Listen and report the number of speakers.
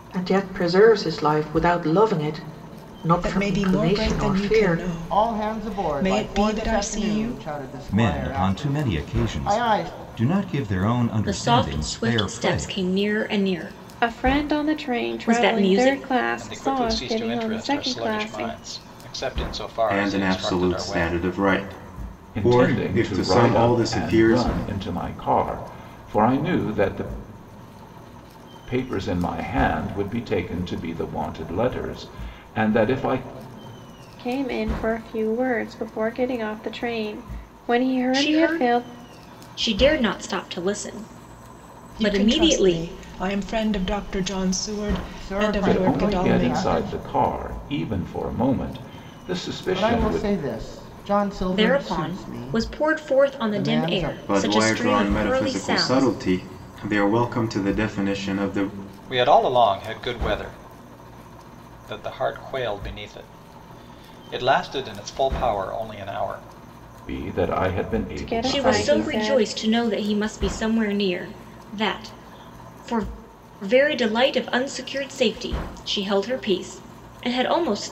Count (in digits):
9